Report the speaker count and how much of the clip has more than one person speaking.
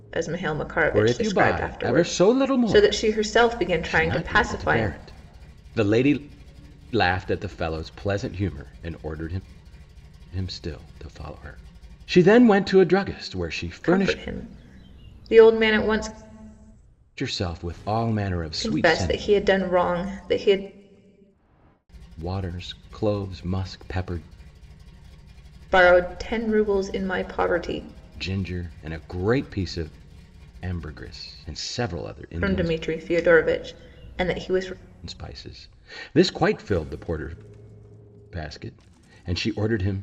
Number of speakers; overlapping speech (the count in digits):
2, about 12%